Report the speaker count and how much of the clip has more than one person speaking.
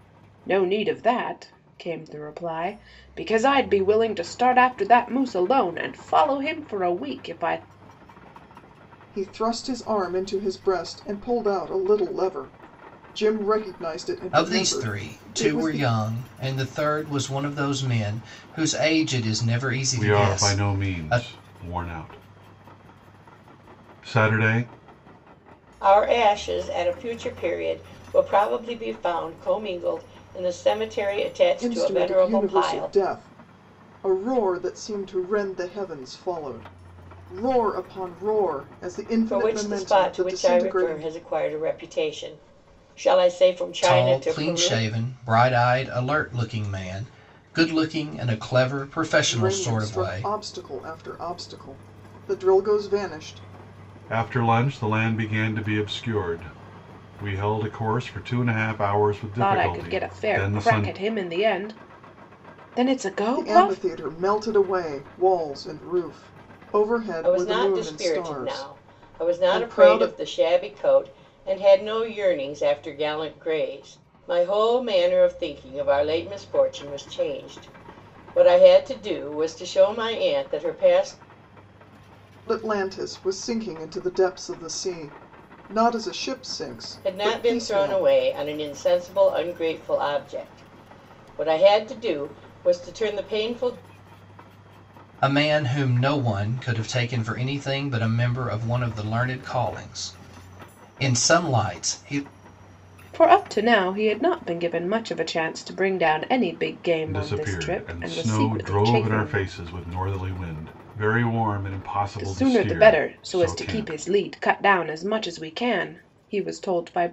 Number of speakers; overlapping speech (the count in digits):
5, about 16%